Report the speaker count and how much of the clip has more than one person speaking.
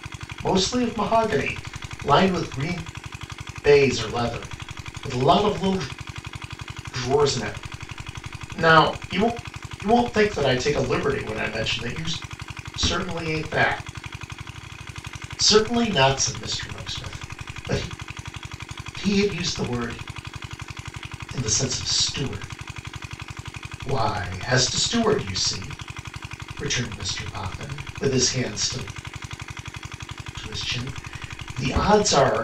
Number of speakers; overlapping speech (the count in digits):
1, no overlap